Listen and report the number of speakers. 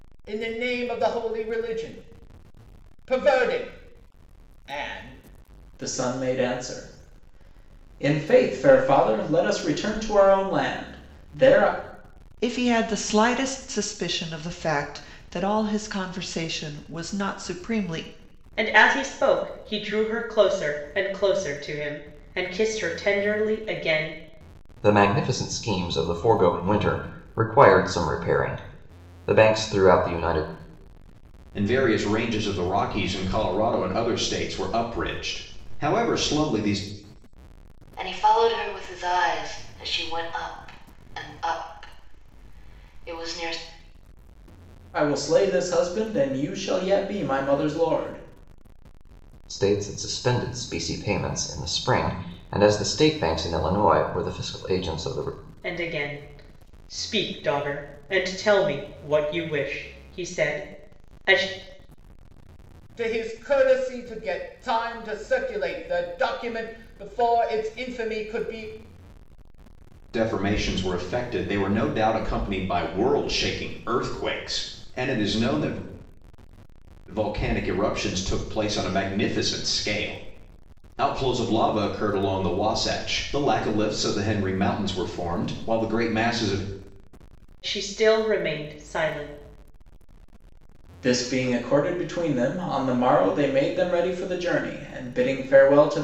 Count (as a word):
seven